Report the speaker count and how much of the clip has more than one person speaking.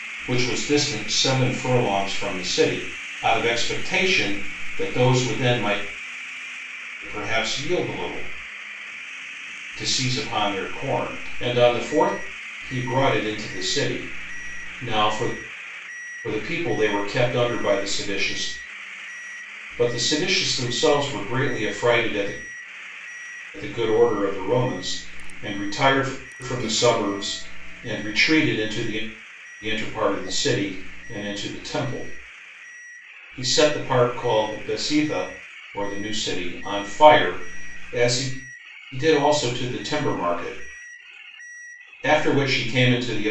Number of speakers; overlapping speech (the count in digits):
1, no overlap